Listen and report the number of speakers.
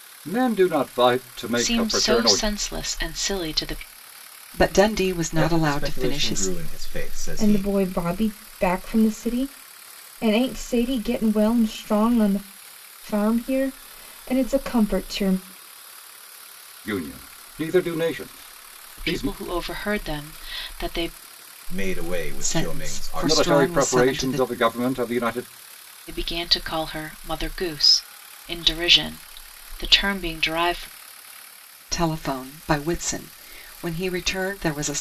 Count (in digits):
5